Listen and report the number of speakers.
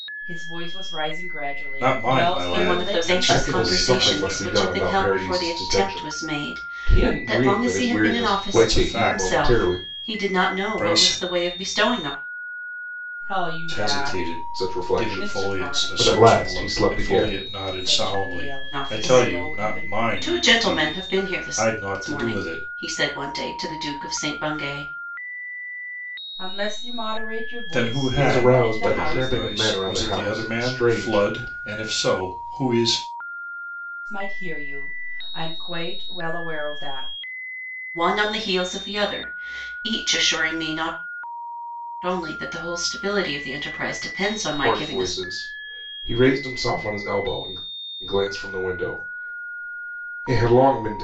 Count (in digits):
4